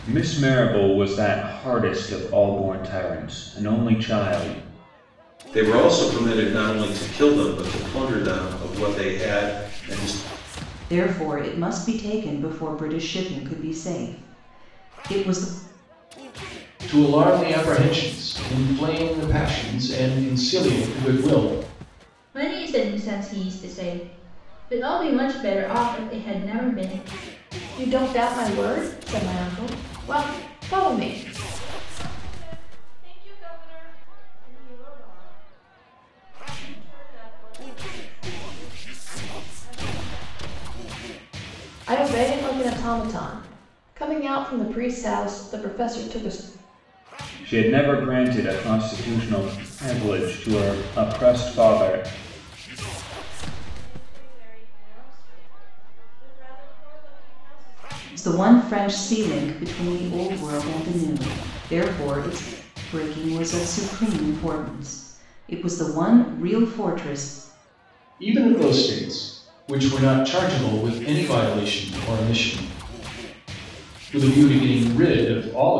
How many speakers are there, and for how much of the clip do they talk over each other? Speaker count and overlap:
7, no overlap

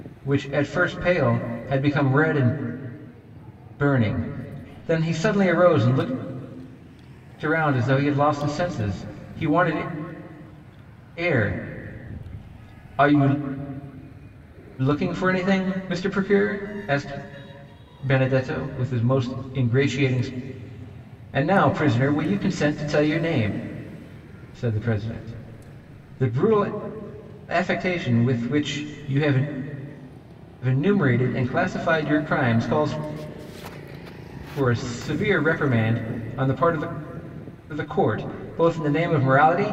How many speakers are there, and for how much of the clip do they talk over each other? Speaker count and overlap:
1, no overlap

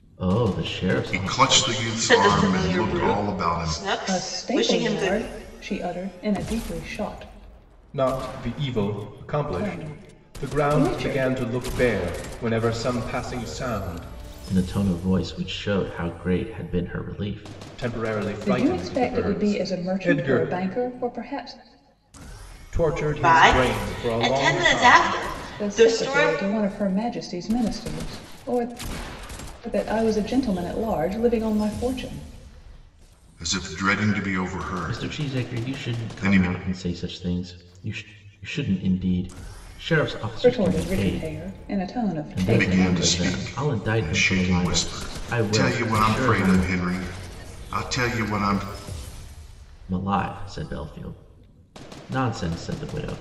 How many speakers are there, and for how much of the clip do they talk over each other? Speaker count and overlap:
5, about 33%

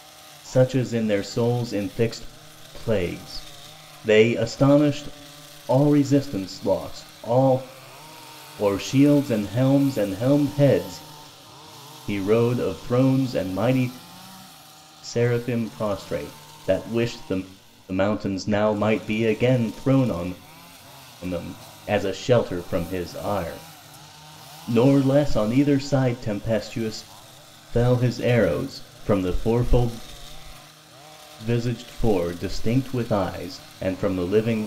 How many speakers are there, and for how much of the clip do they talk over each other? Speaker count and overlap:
1, no overlap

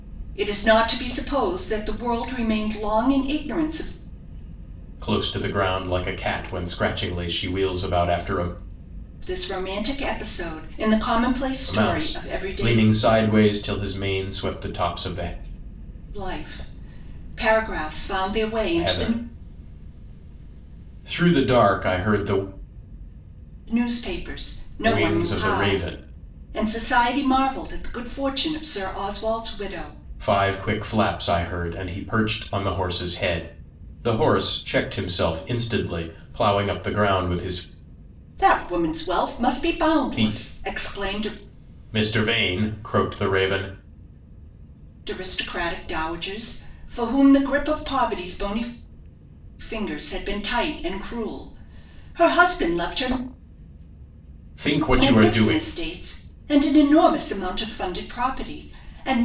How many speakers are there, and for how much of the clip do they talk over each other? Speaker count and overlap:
2, about 8%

